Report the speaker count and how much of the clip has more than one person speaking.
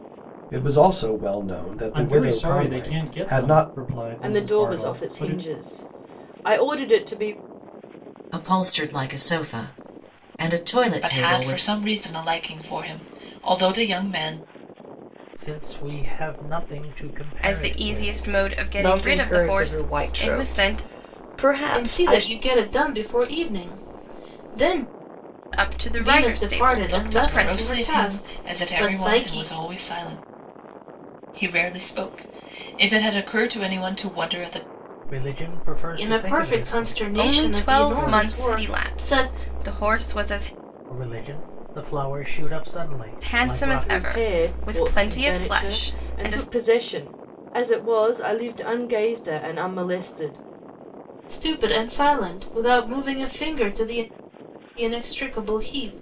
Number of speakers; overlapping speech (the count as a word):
nine, about 31%